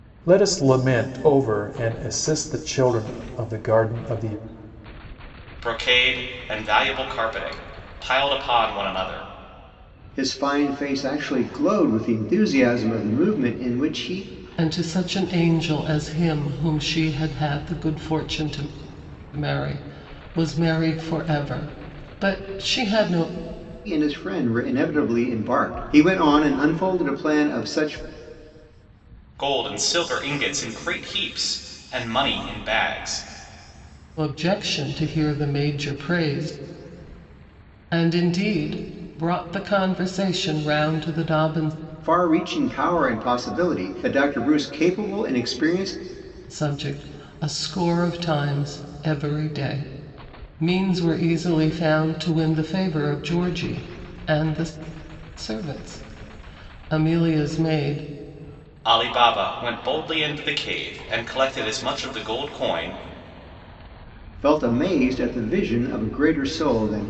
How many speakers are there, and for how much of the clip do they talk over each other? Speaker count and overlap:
four, no overlap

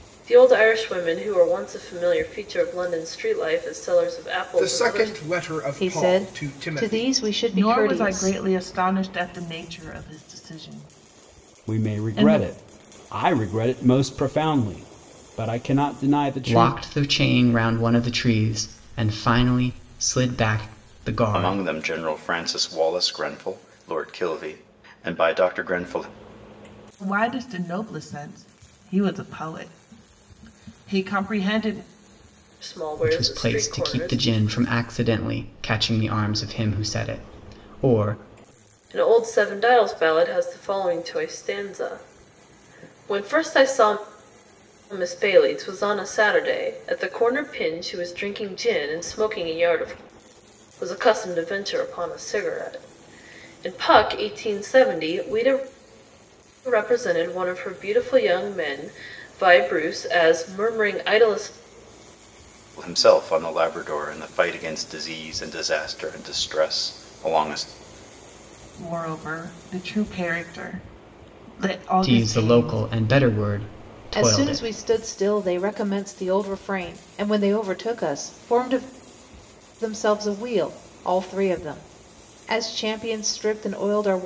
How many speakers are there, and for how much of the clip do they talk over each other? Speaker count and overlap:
seven, about 9%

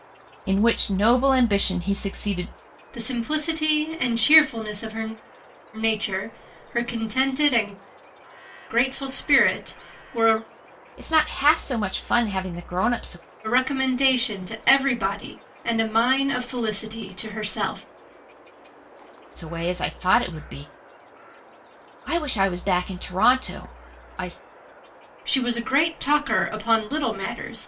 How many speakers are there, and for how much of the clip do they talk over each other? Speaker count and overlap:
two, no overlap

